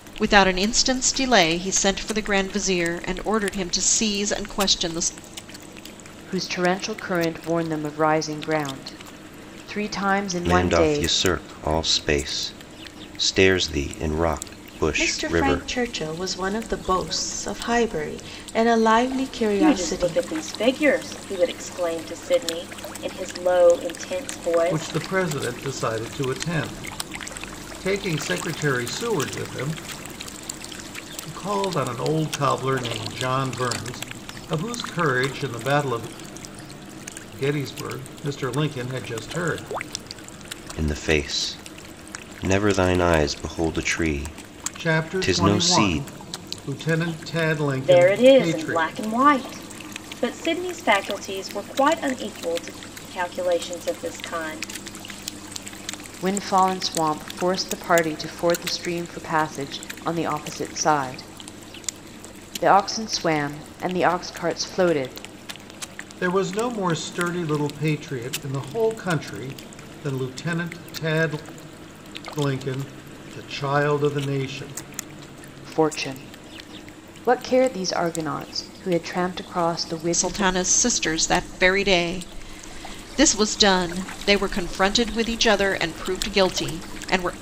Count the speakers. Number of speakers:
six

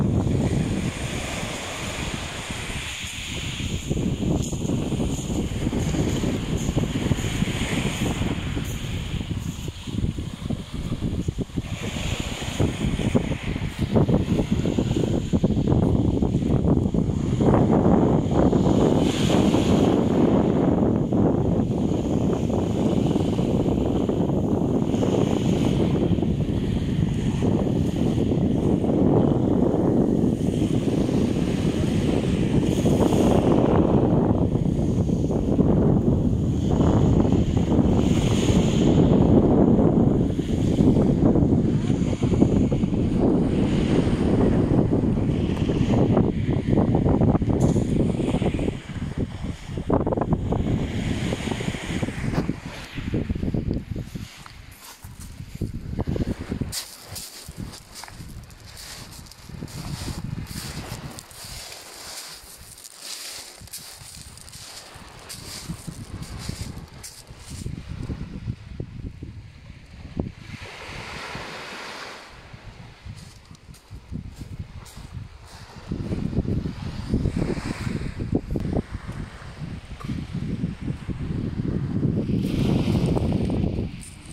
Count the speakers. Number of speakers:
zero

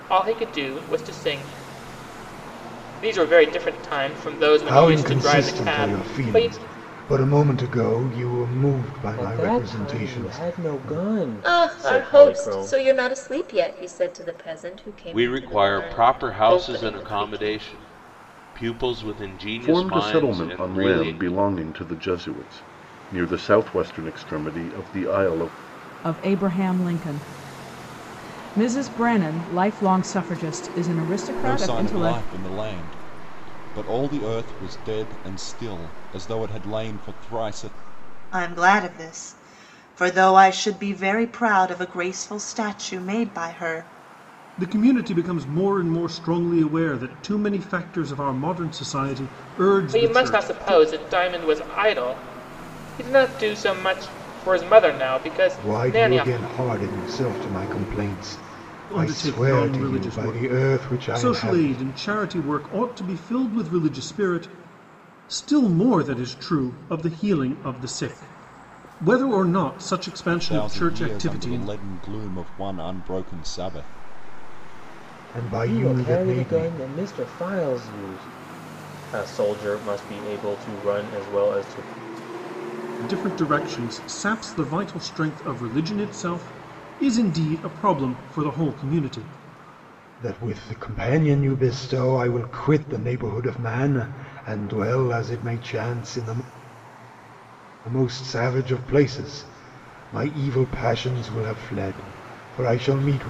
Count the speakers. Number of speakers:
ten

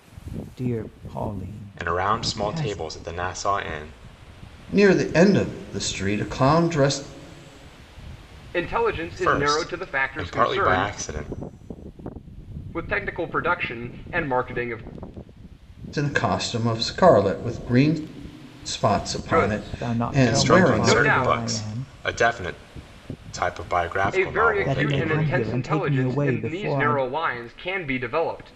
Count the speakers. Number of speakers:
four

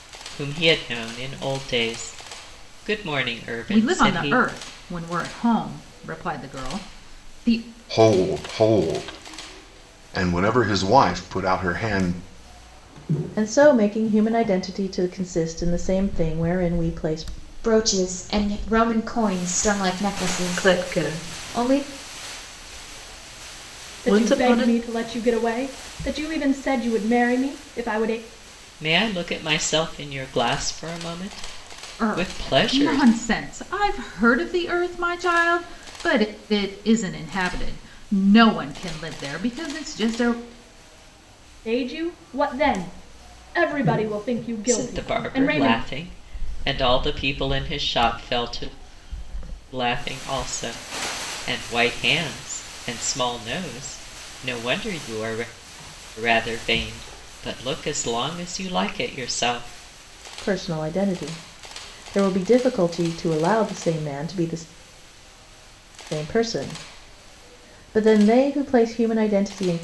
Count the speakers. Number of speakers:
seven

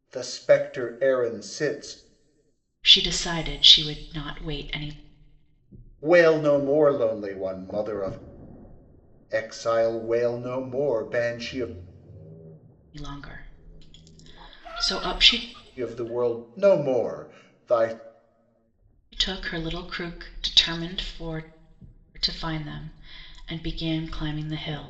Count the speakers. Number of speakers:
two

